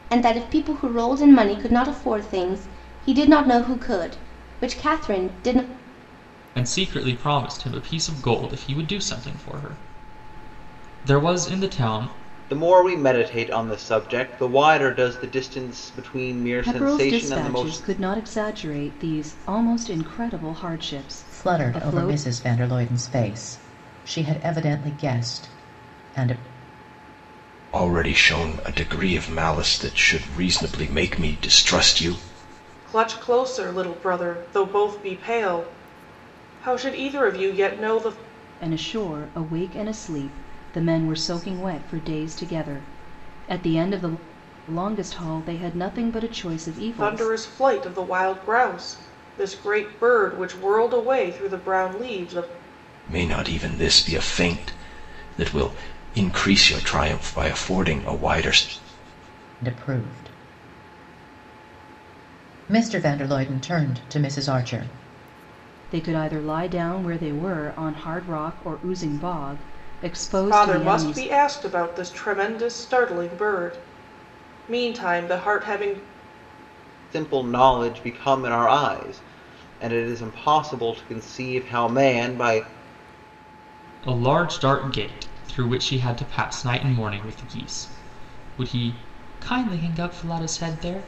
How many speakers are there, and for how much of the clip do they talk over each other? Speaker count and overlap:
7, about 4%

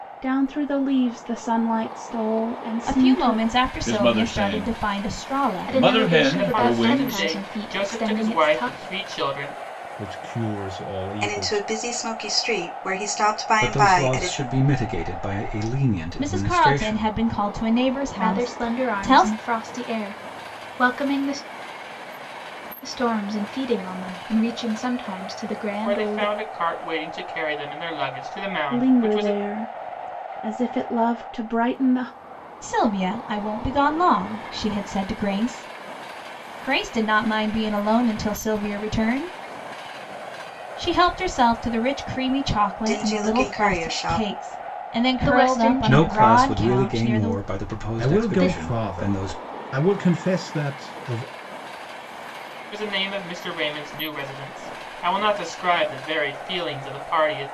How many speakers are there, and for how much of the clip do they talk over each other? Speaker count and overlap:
8, about 28%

